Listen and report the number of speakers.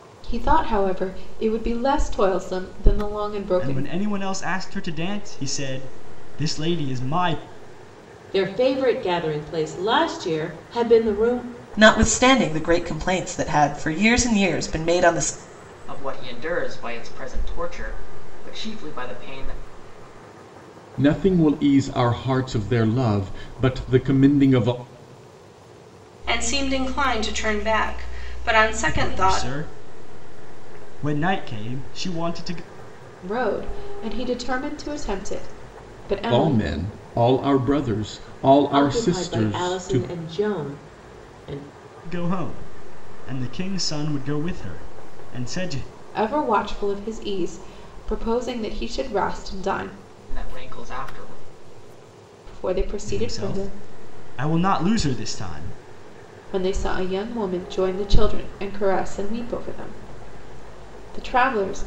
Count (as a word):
seven